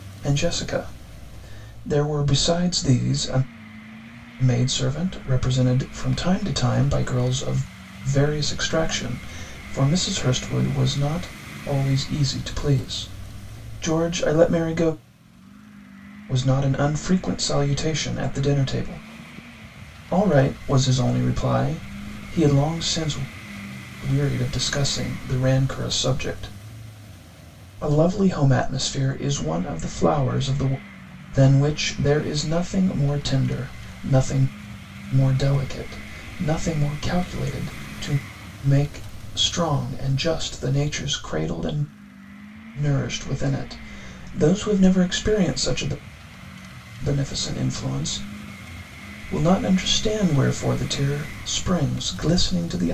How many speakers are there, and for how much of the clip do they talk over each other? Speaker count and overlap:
1, no overlap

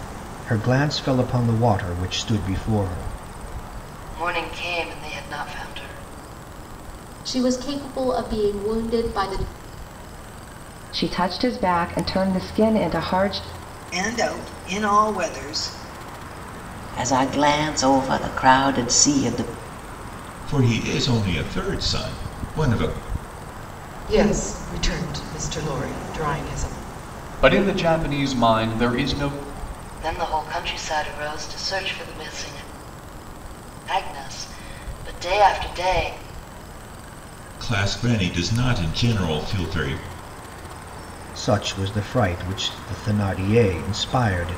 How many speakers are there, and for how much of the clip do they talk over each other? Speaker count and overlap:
9, no overlap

